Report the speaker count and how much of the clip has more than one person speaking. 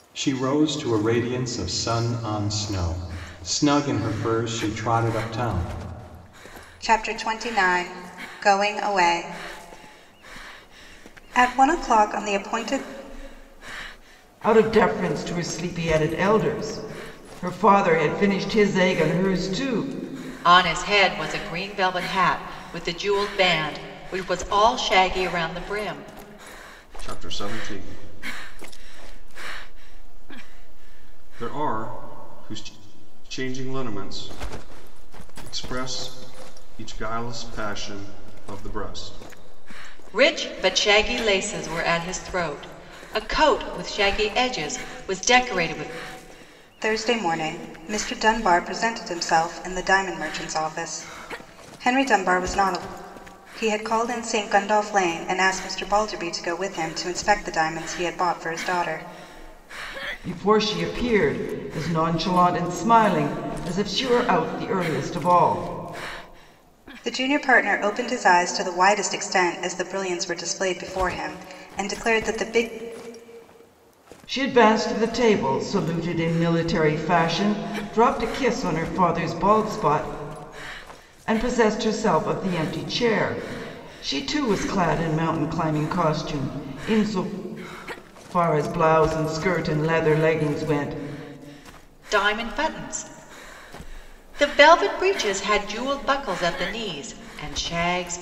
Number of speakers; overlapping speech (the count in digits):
5, no overlap